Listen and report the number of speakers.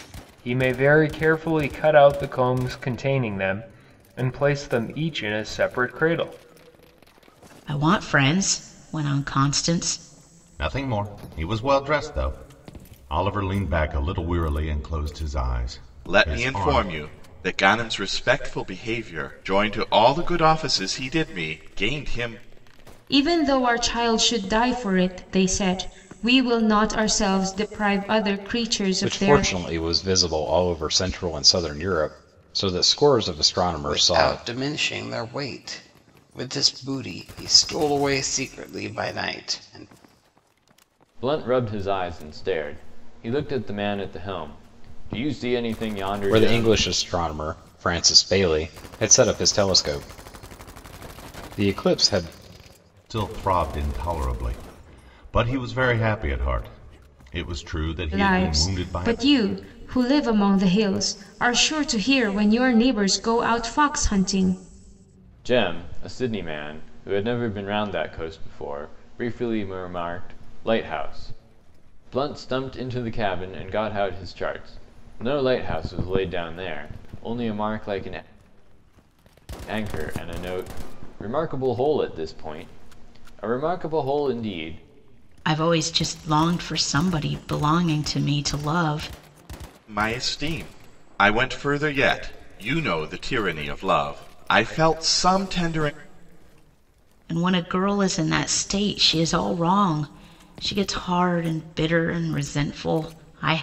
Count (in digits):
8